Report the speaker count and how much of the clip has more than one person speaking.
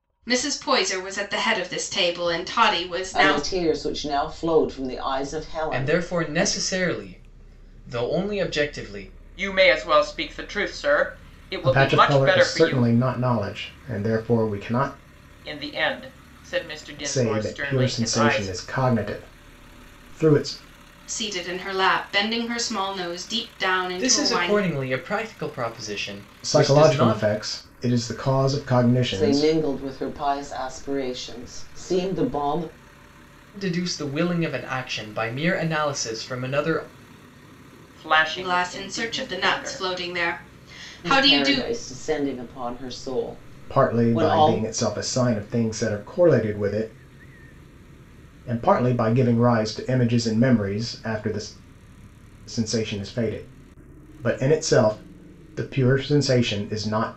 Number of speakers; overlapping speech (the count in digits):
5, about 16%